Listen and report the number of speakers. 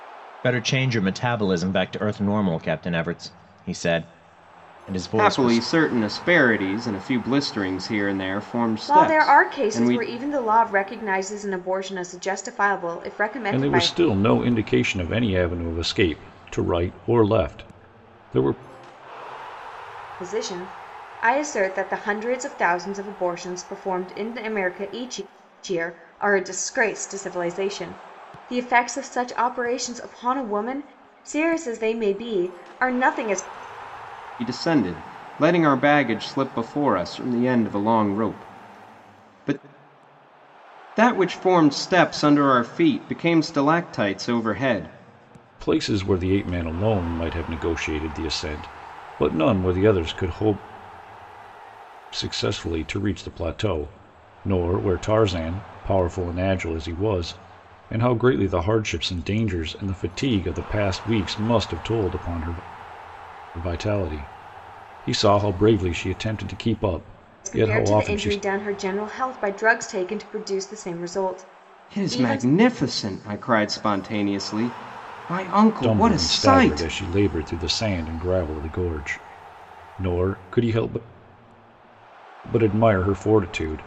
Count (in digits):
4